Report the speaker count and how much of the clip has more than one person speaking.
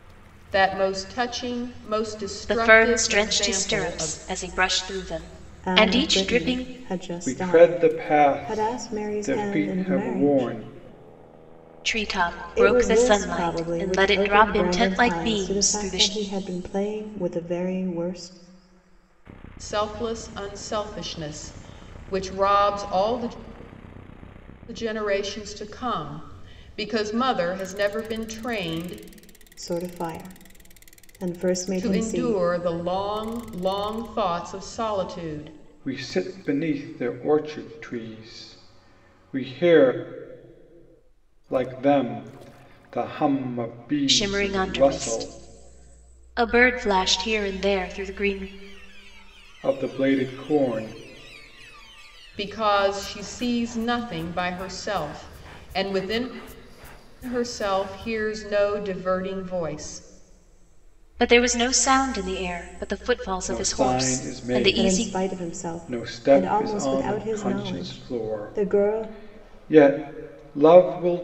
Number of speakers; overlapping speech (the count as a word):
four, about 26%